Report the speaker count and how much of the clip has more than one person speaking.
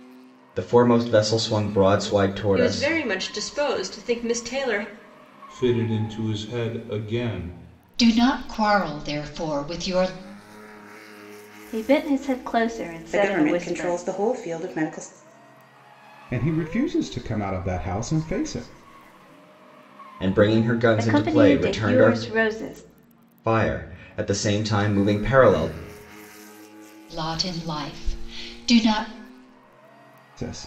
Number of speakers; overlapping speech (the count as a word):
seven, about 9%